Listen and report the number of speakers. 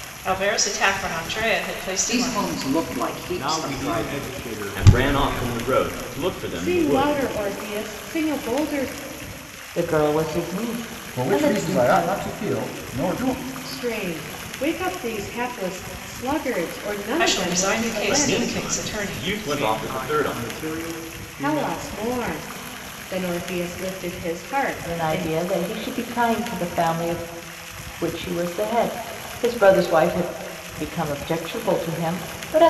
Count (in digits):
7